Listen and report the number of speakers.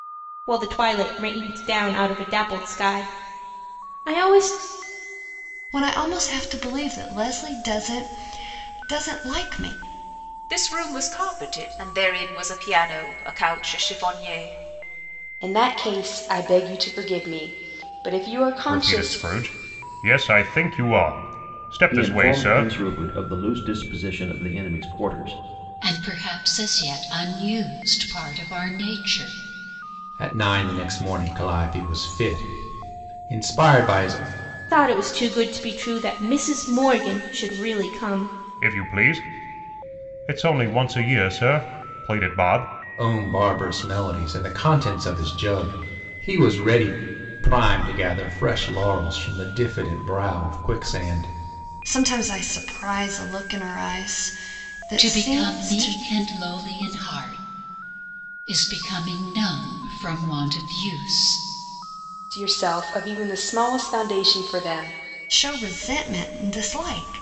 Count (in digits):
8